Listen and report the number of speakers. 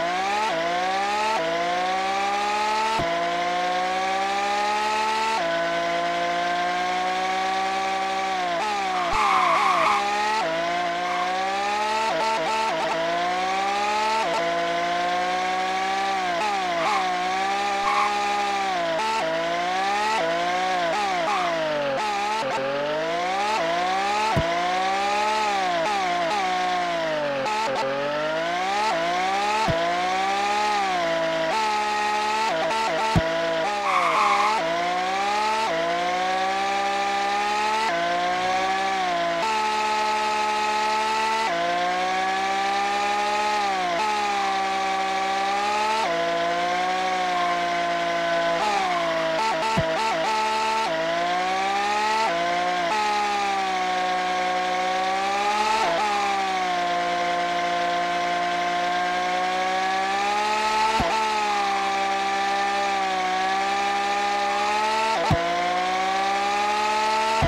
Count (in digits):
0